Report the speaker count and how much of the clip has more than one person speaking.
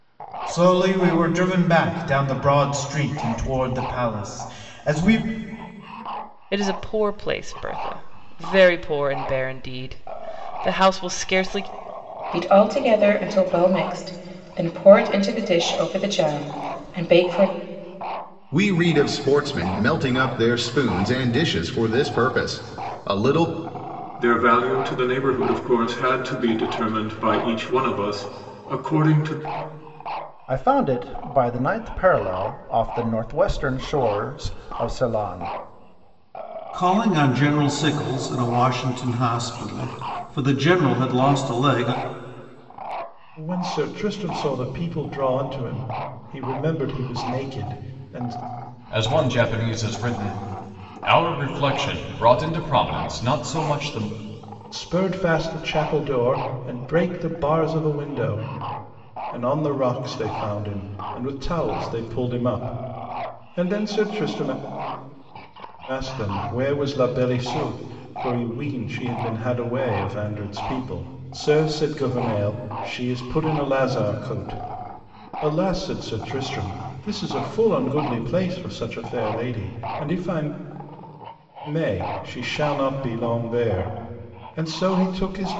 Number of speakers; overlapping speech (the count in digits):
9, no overlap